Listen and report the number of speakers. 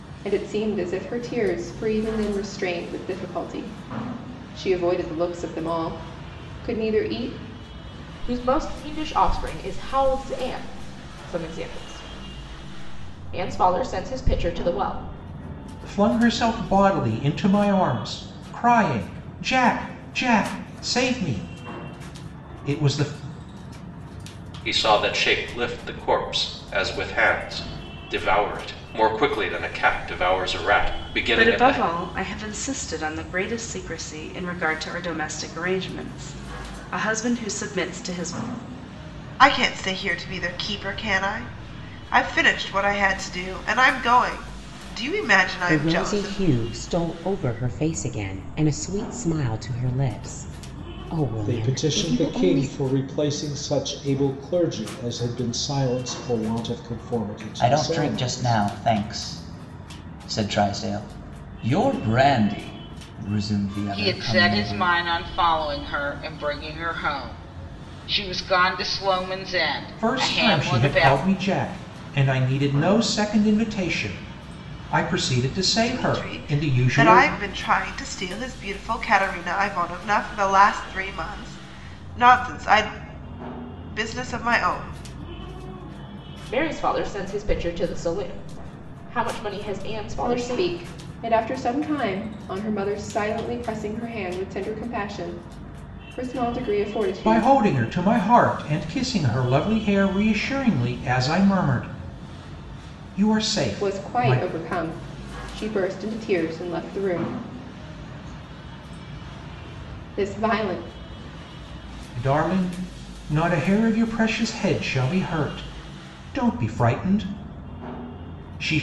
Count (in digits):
10